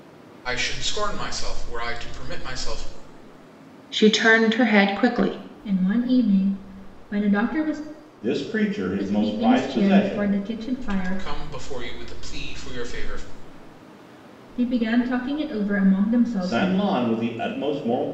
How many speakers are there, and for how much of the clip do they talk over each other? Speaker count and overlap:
4, about 12%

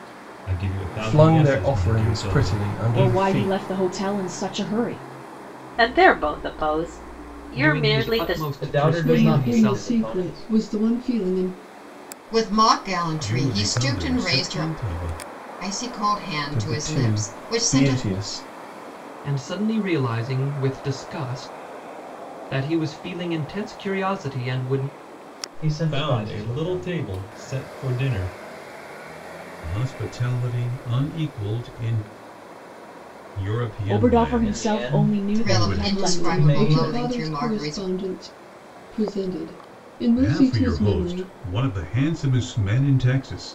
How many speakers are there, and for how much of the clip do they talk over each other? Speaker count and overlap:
9, about 34%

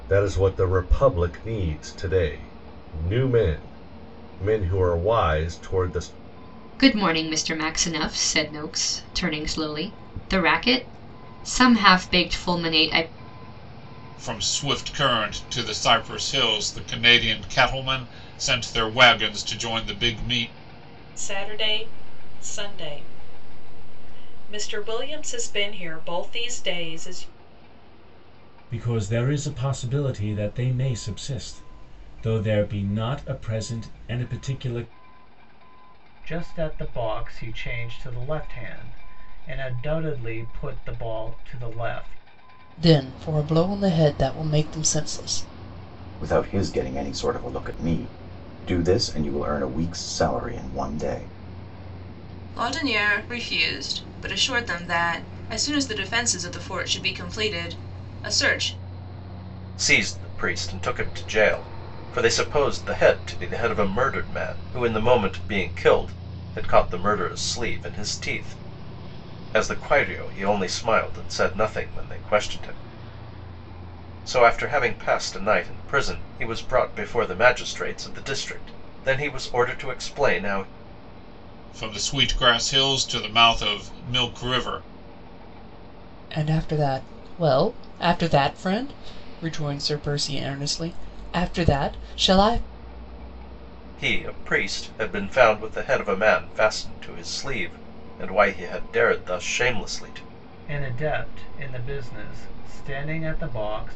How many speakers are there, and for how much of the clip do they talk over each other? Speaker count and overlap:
10, no overlap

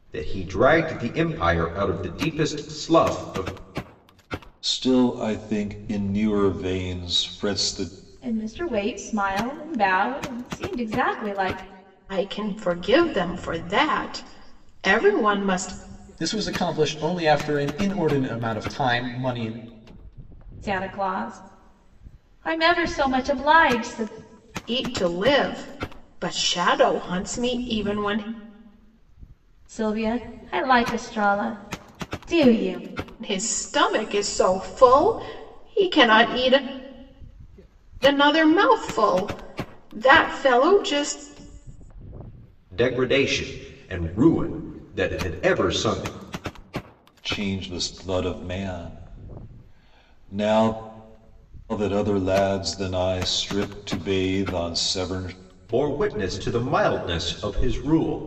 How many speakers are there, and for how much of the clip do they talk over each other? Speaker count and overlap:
5, no overlap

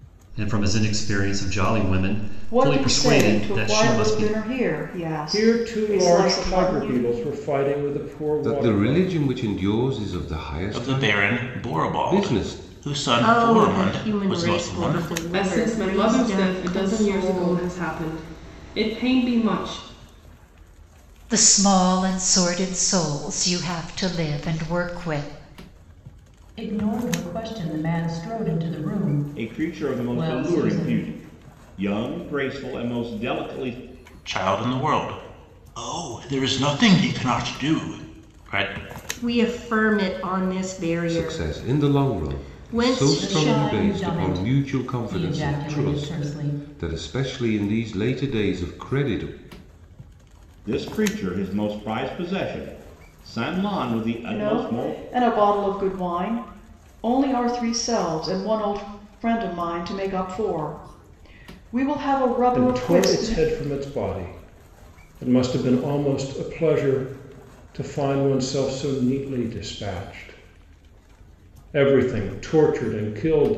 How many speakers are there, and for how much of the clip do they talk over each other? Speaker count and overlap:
10, about 27%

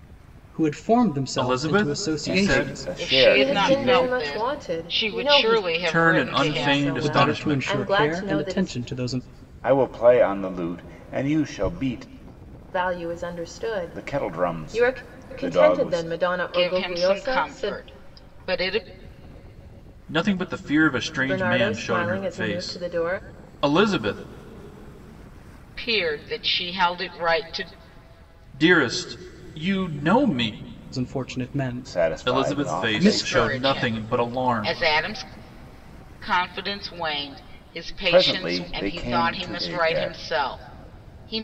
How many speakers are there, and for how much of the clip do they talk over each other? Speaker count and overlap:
5, about 42%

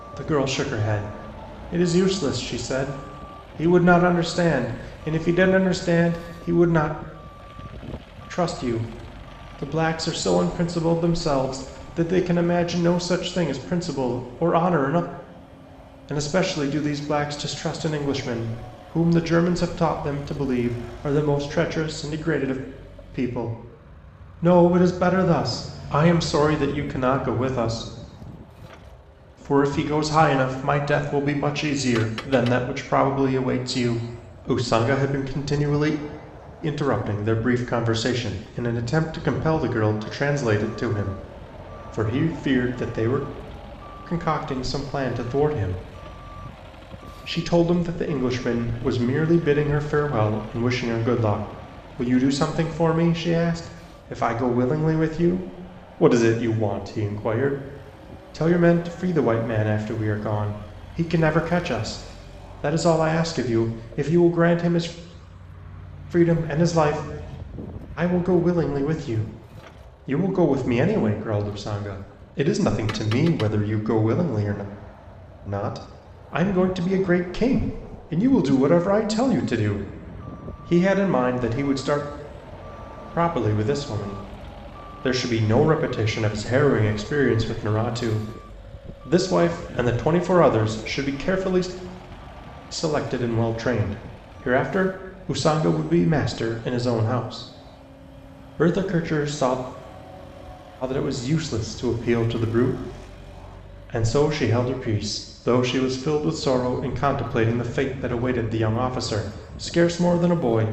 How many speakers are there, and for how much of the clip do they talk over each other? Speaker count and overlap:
1, no overlap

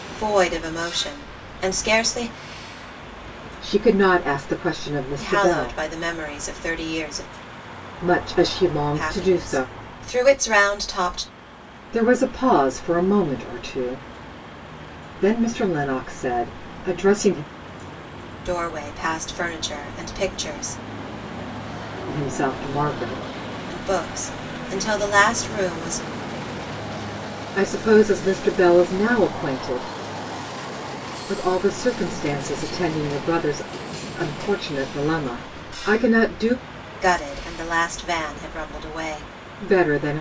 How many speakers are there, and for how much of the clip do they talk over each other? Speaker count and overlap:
2, about 3%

